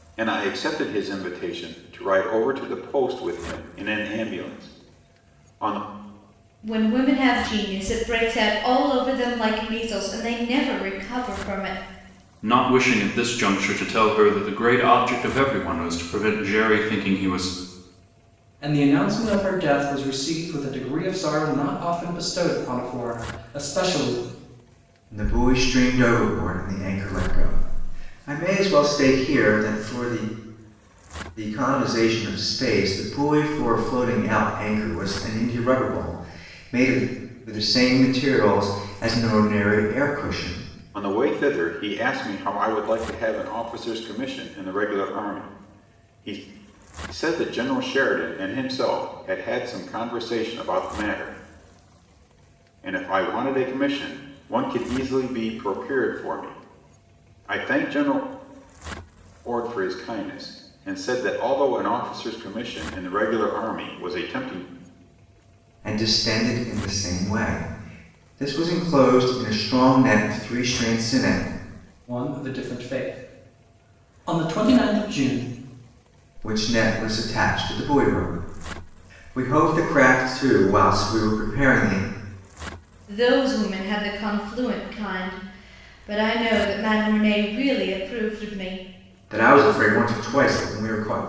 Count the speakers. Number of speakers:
five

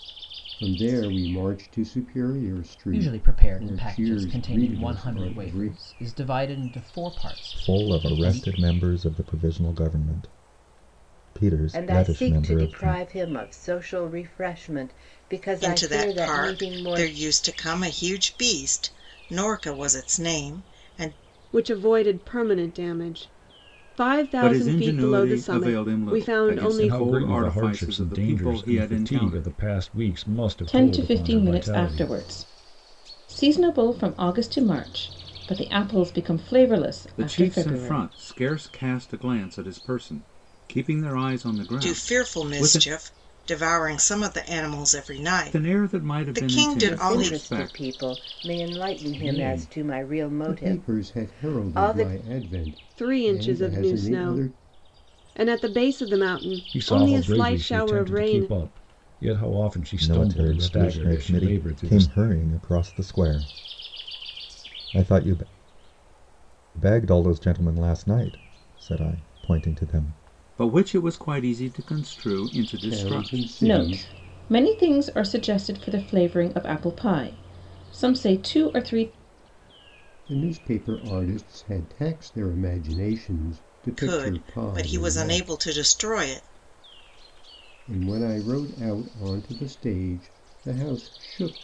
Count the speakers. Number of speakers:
nine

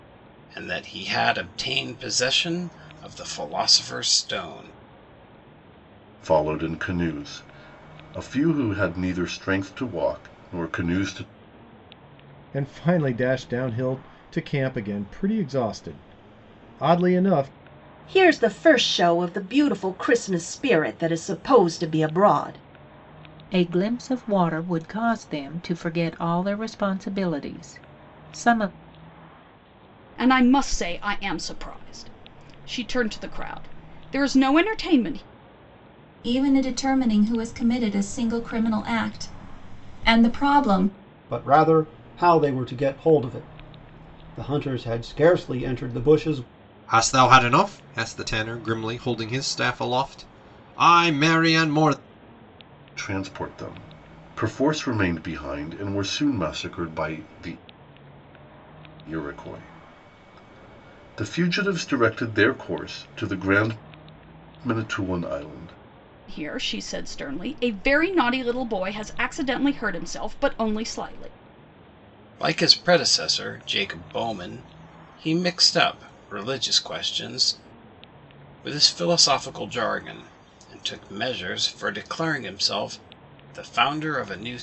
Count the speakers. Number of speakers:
nine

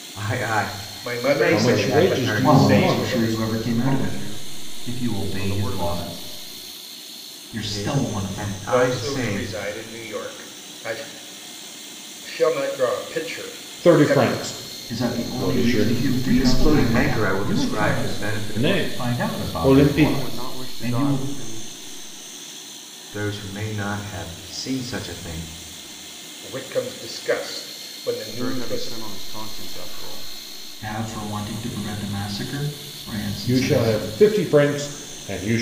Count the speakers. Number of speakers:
six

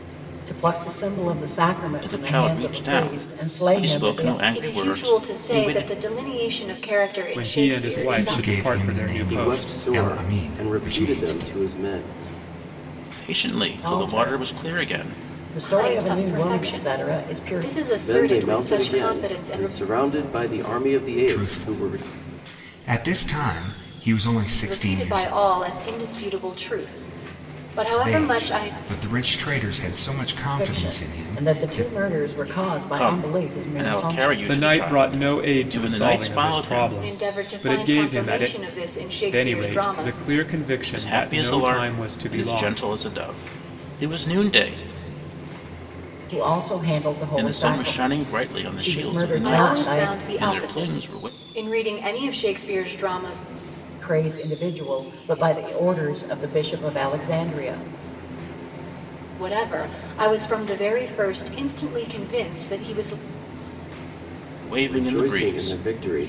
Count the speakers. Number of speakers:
six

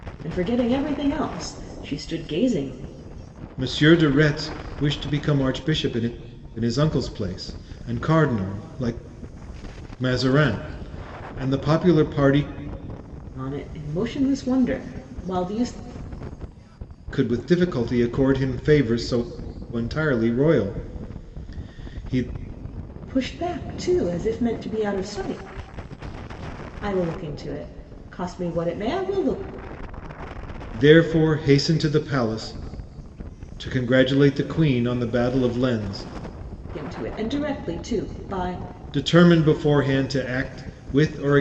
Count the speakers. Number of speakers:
two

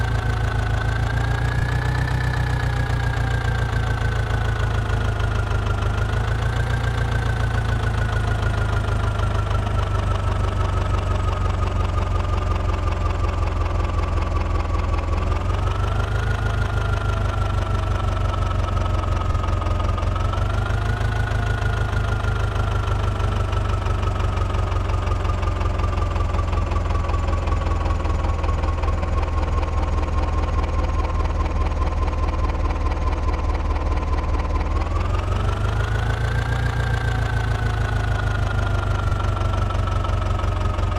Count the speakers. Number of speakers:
zero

